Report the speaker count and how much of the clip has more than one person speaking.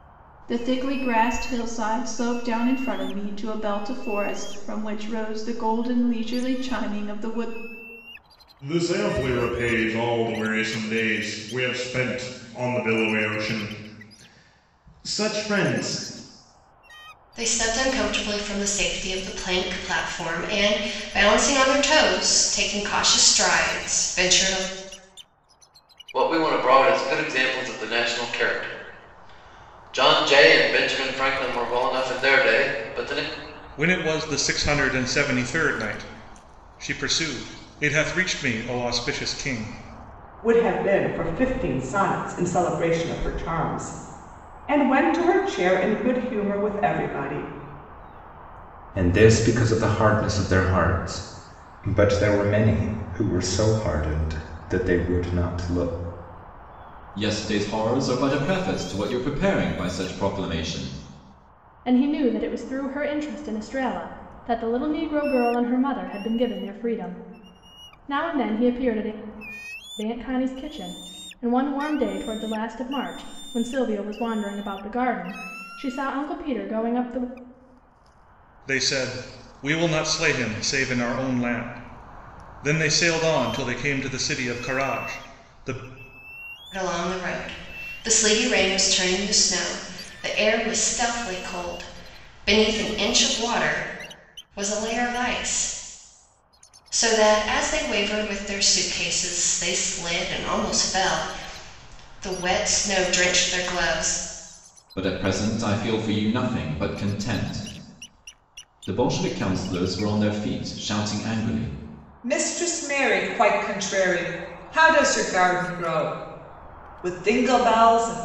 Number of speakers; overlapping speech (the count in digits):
9, no overlap